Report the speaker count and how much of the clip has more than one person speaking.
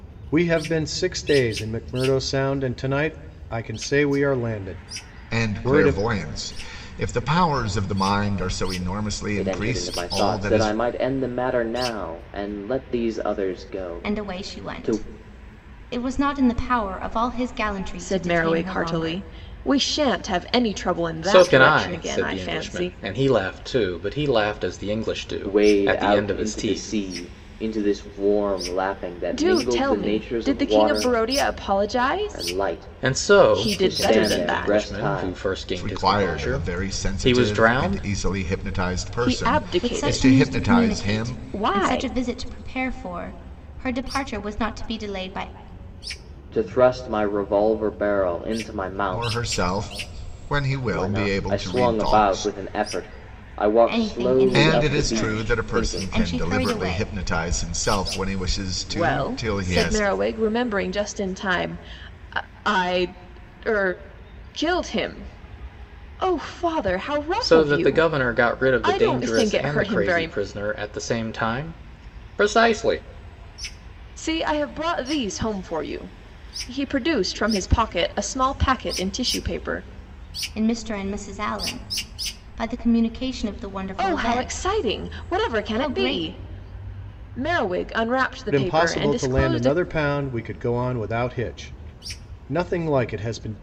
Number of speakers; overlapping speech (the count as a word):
six, about 34%